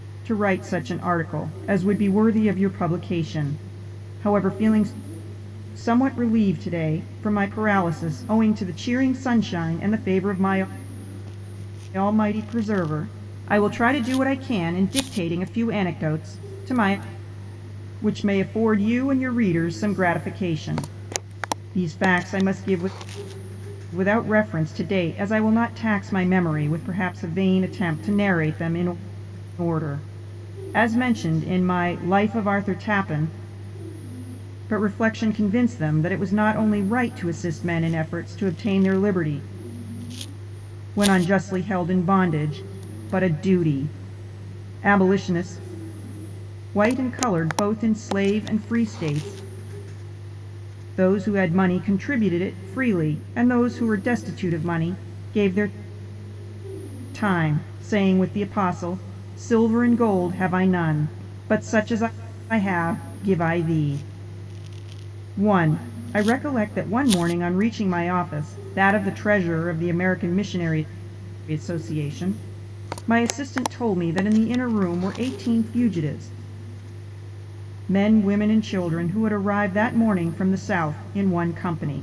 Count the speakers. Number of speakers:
1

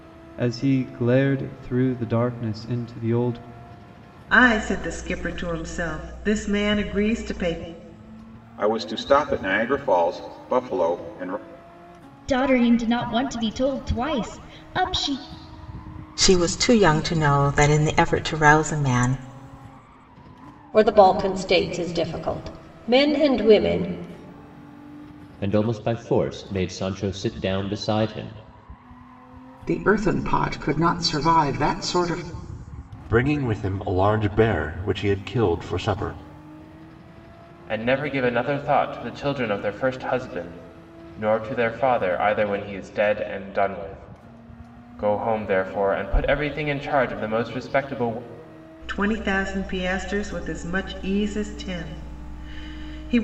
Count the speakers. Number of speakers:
10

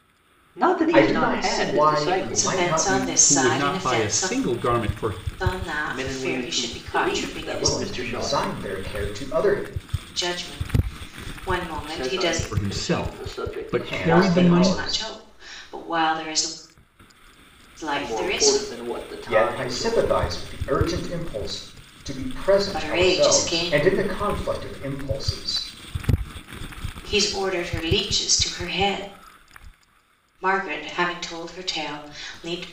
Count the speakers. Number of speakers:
4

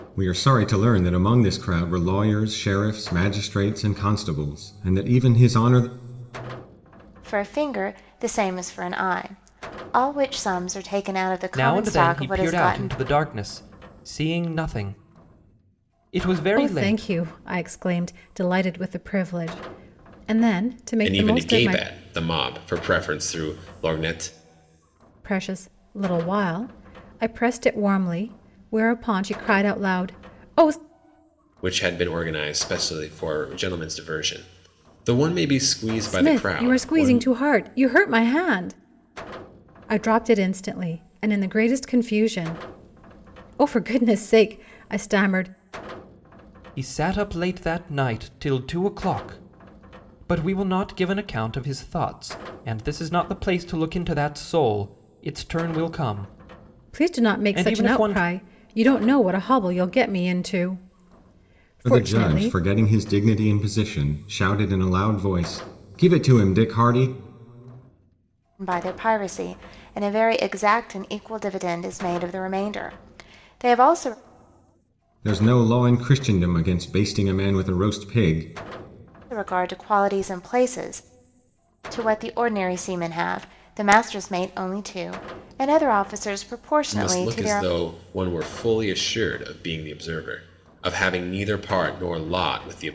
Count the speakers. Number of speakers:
5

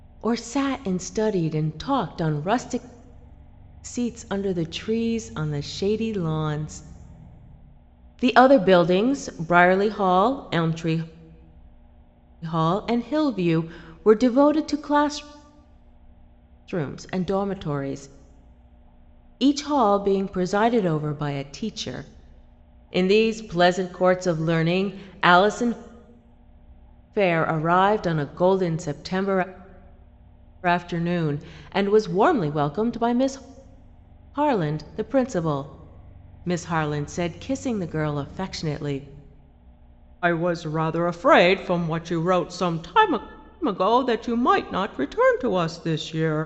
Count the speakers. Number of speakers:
1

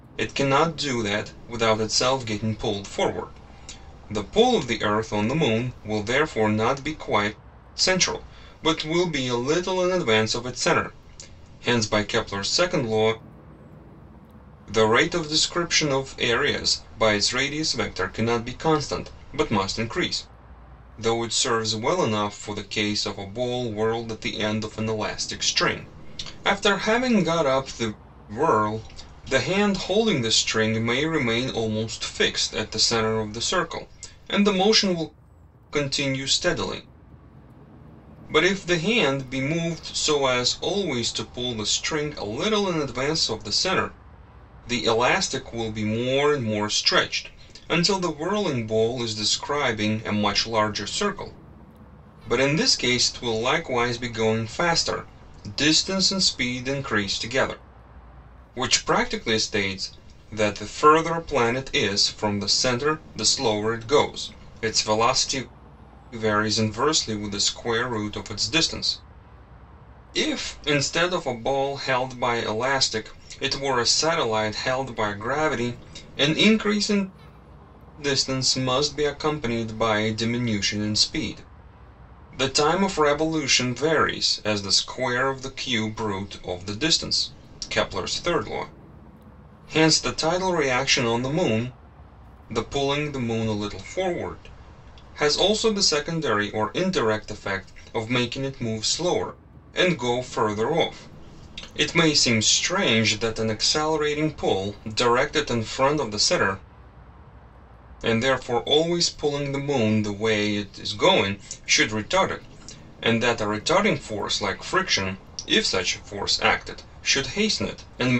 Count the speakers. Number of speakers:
1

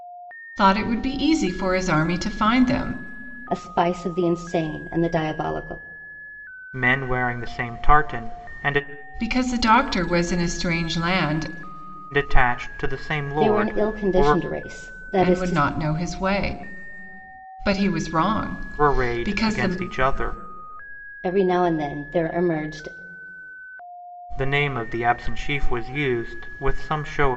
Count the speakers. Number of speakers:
3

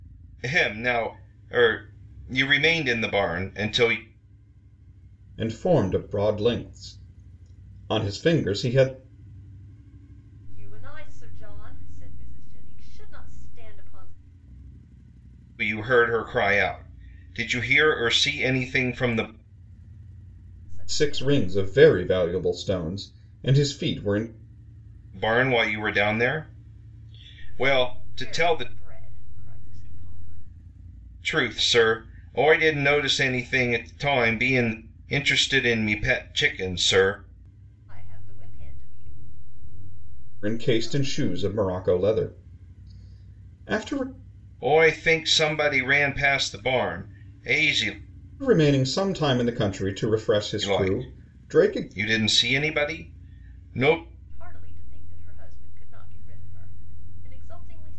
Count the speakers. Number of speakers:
3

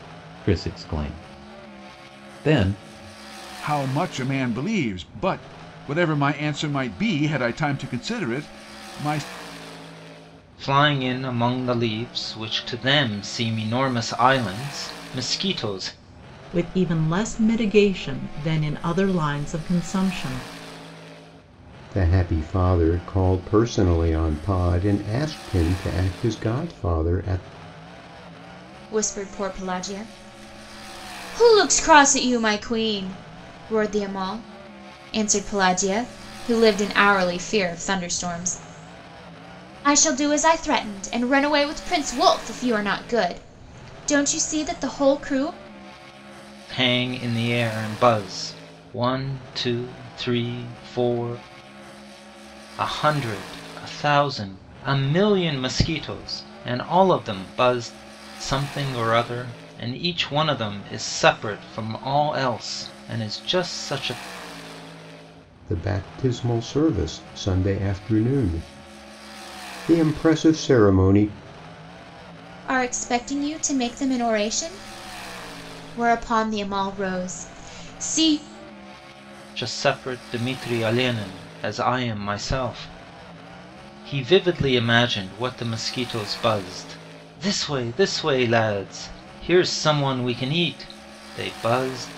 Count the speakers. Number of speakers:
6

